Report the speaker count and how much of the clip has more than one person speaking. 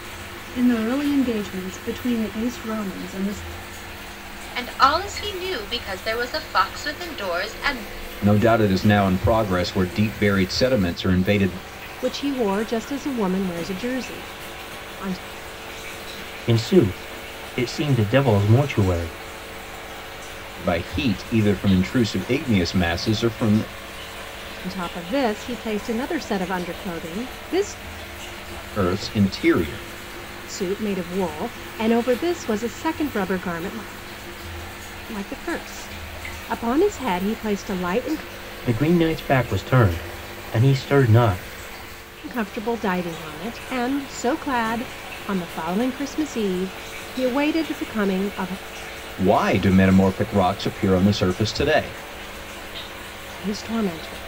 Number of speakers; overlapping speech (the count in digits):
5, no overlap